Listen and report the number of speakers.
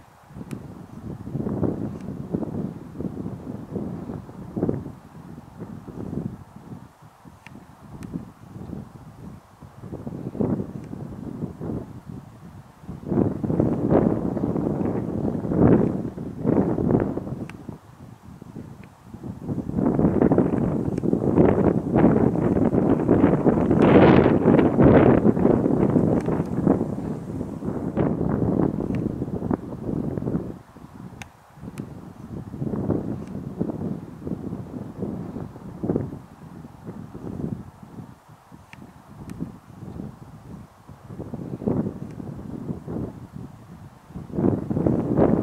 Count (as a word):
zero